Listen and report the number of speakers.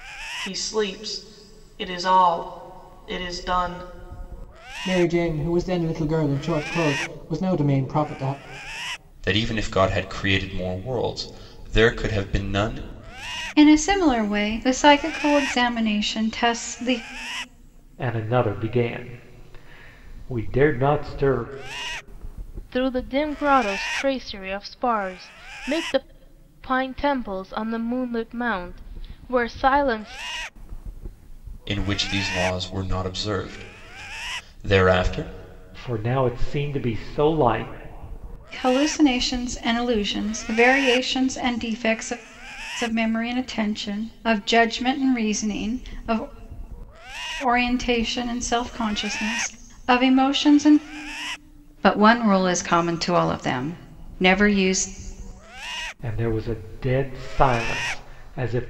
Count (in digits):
6